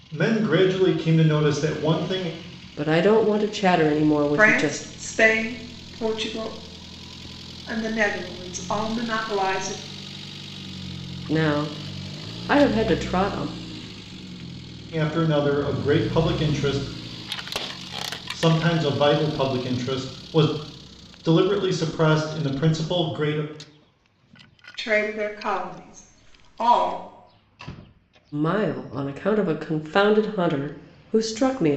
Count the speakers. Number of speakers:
three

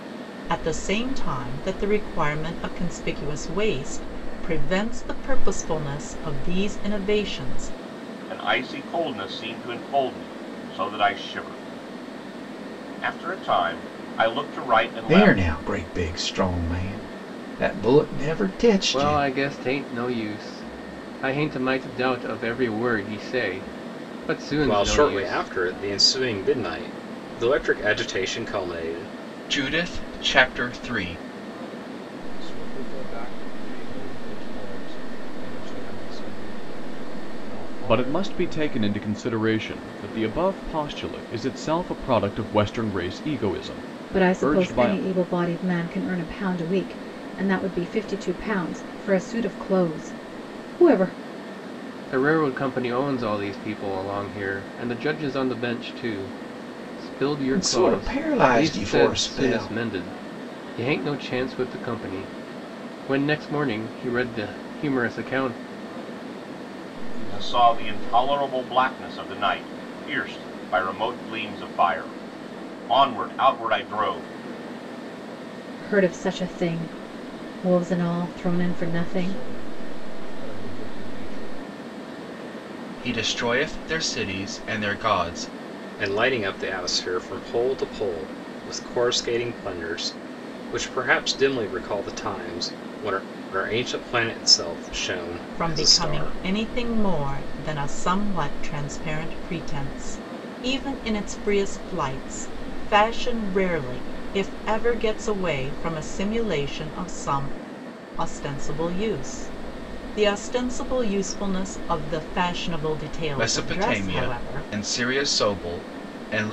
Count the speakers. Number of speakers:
nine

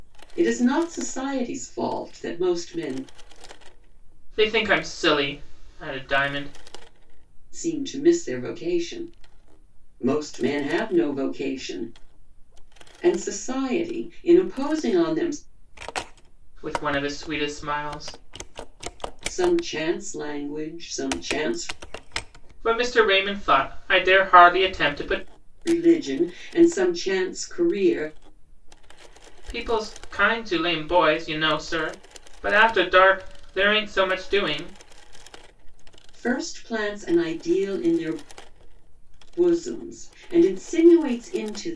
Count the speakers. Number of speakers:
two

